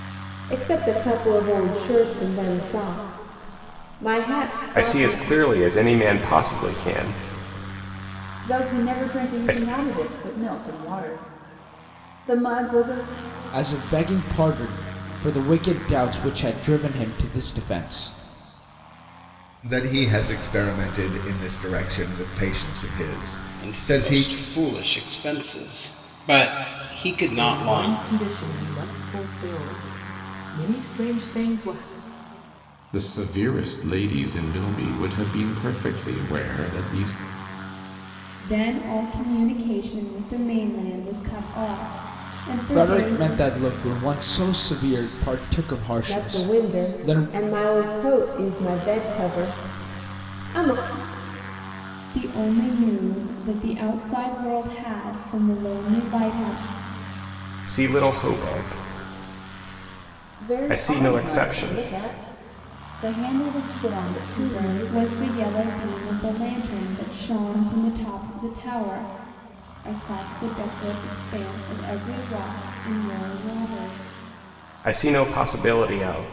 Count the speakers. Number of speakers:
nine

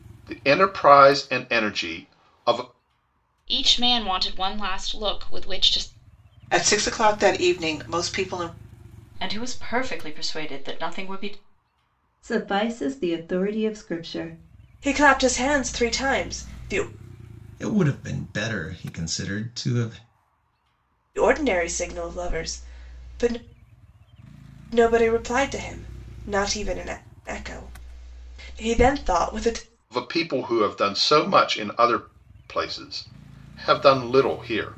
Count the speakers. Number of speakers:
seven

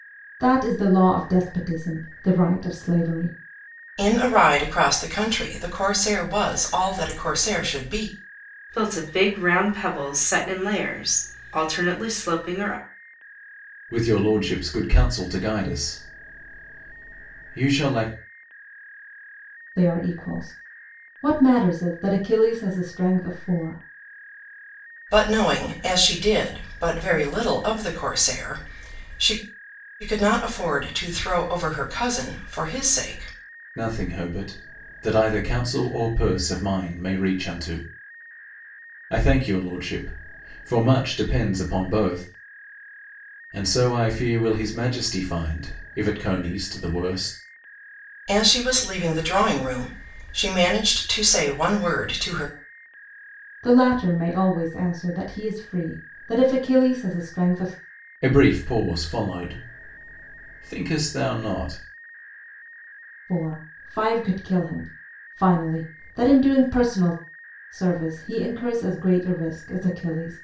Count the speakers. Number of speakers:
four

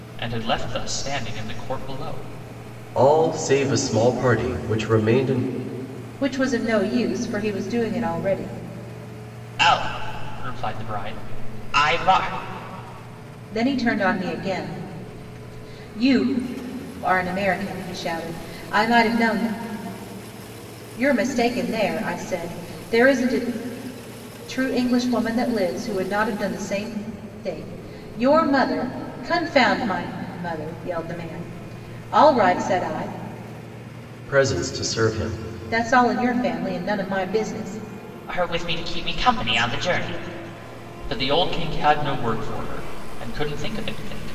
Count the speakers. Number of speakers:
three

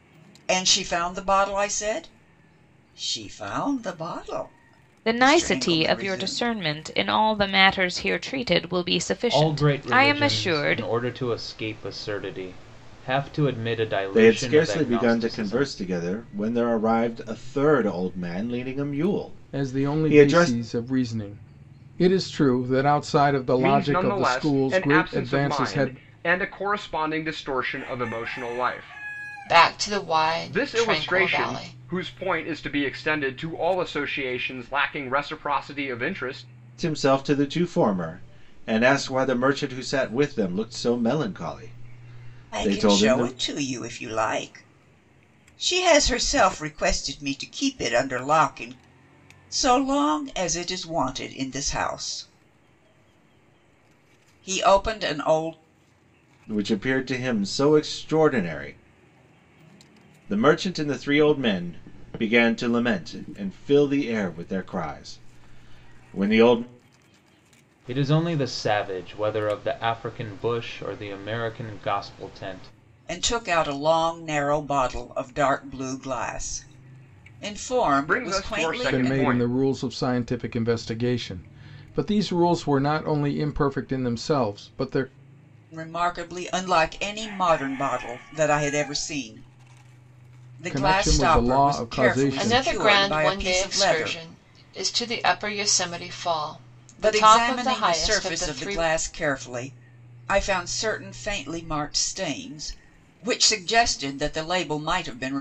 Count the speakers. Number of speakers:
seven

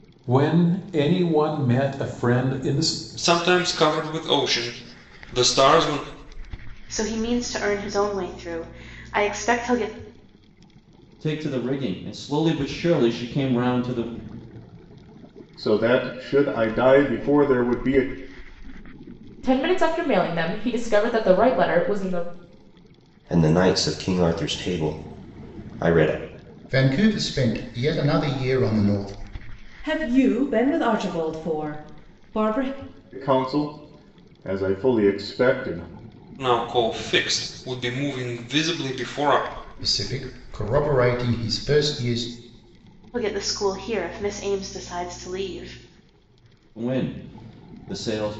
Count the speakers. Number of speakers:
nine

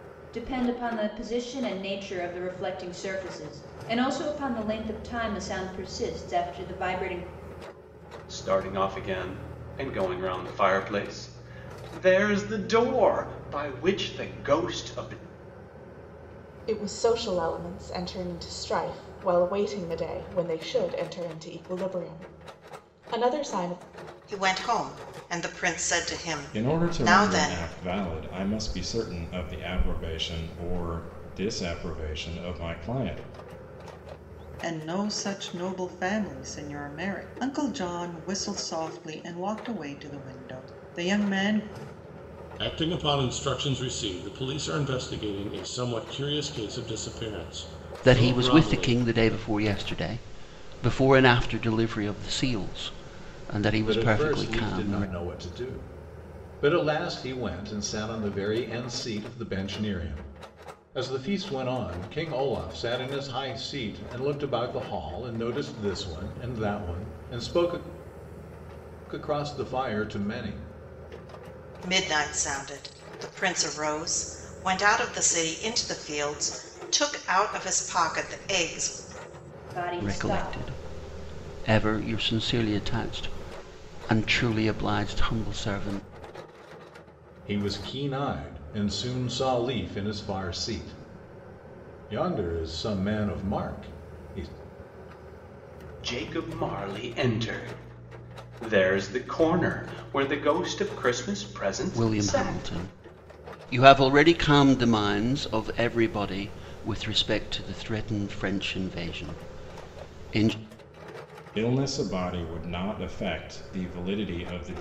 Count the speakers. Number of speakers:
nine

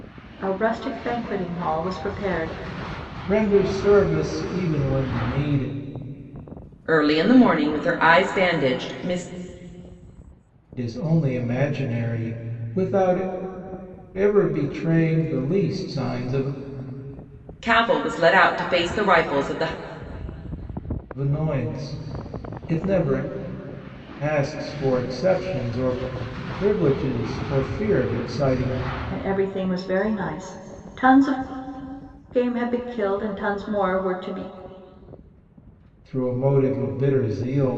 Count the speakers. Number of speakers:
three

